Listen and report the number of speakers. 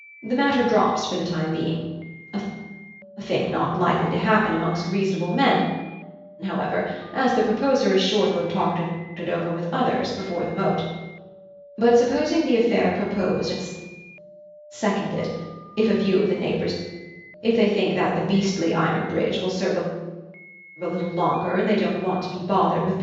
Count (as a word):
one